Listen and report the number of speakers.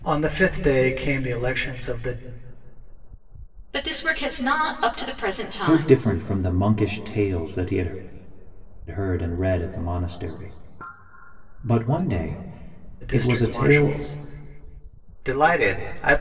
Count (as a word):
three